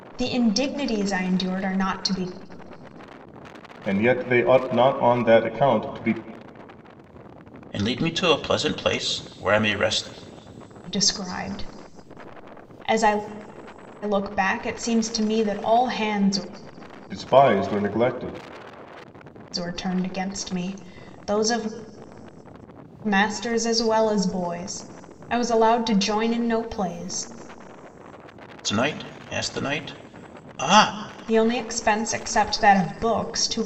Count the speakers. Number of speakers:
3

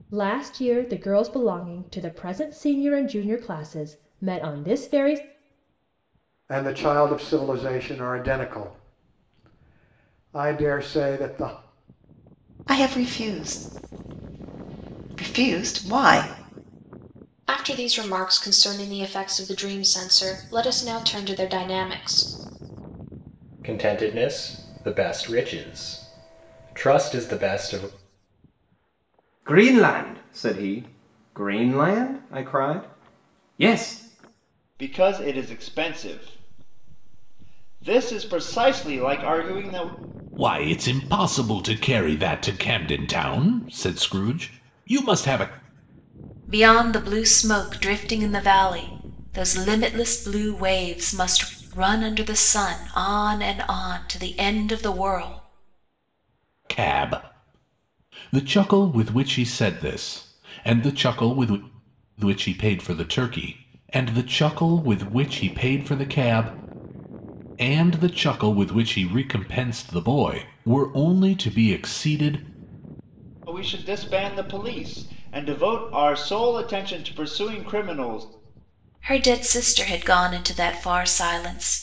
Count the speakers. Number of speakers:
9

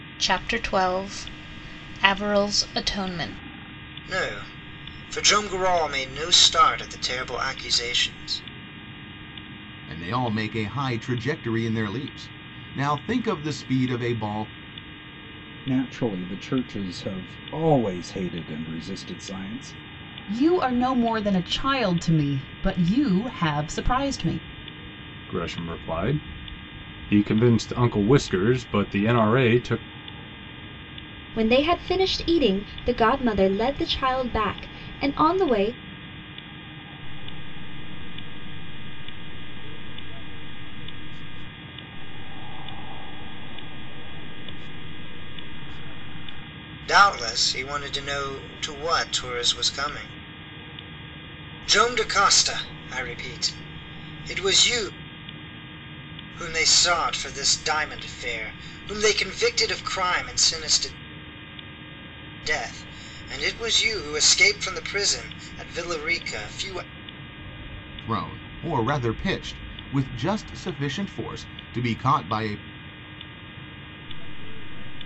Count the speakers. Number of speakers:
8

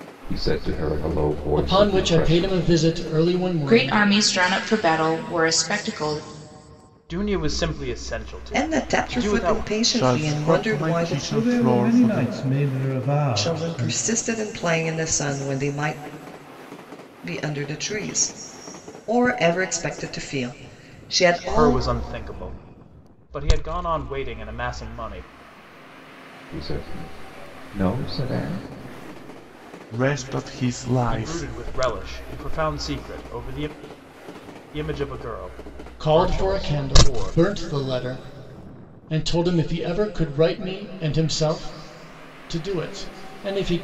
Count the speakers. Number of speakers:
7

